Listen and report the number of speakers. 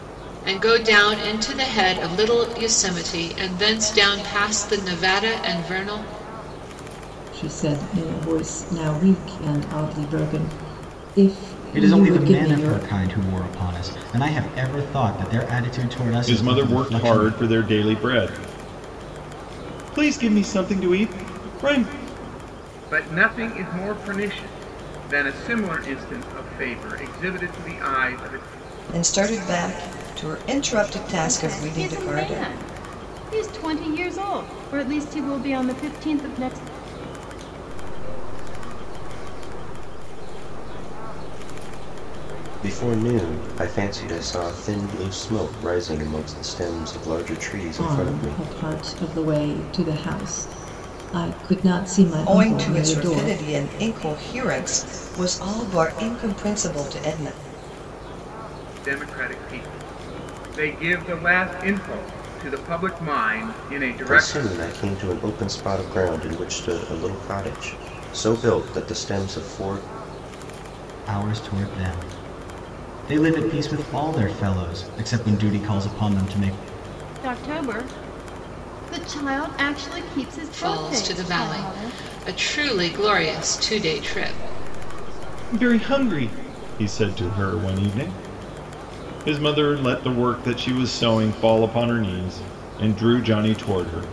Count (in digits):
9